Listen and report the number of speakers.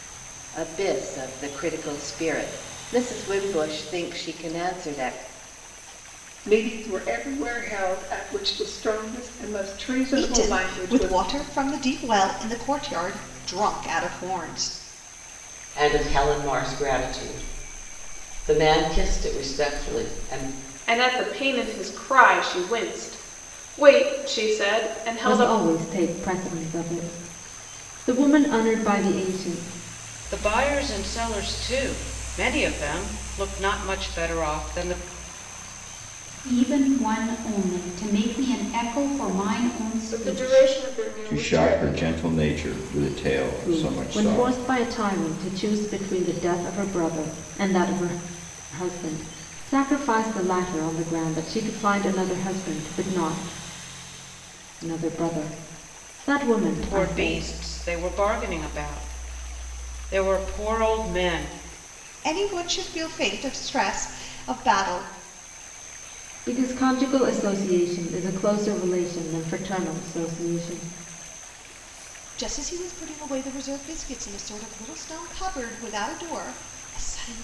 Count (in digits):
10